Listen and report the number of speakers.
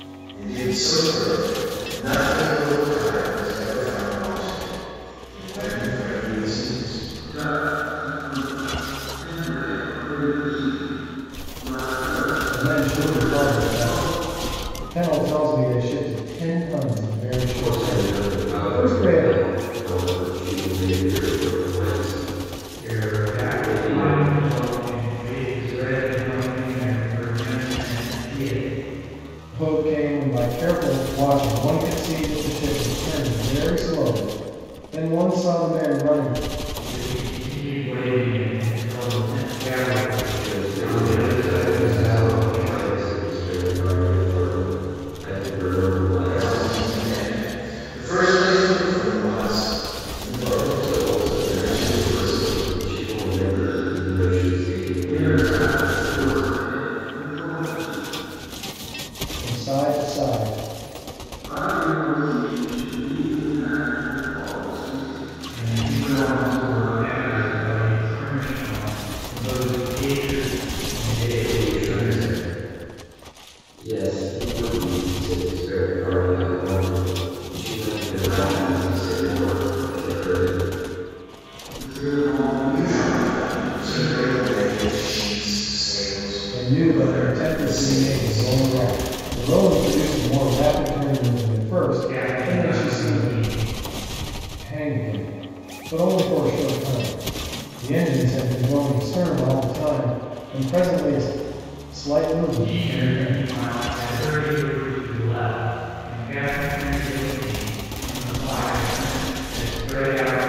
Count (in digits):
5